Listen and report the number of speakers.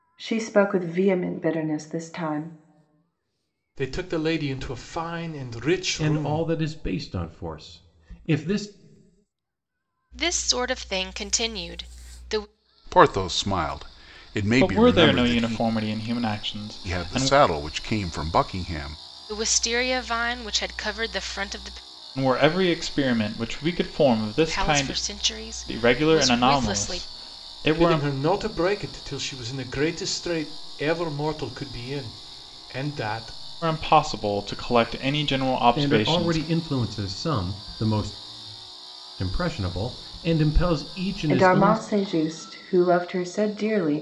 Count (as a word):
six